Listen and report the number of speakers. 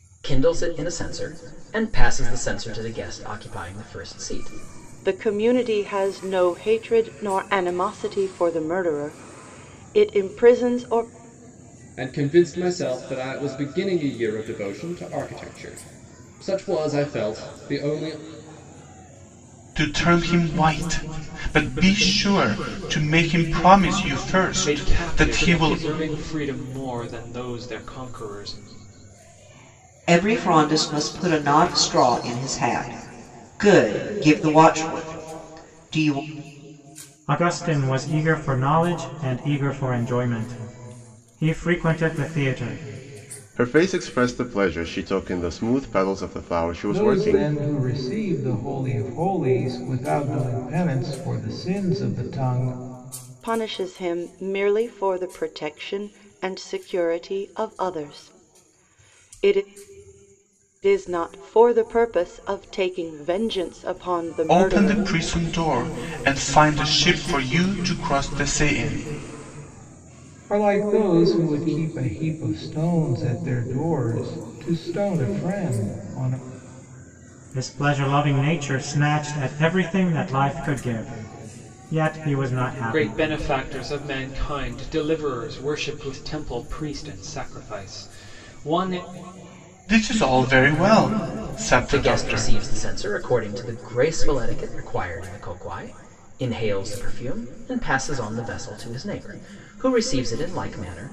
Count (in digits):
9